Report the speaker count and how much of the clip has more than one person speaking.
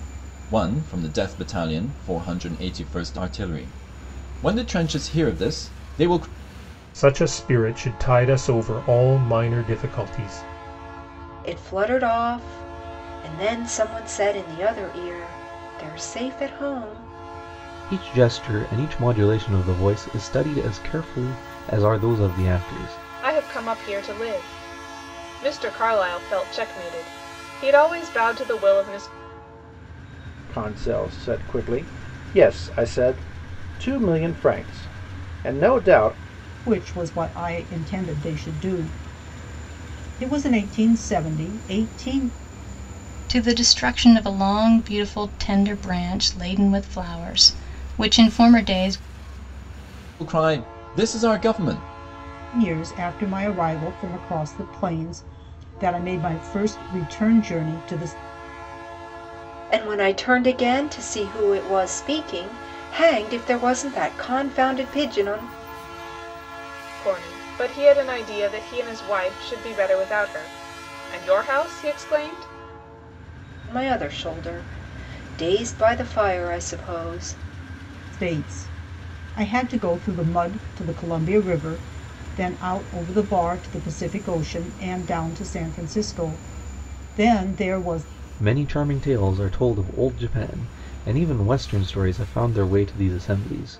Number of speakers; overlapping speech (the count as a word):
eight, no overlap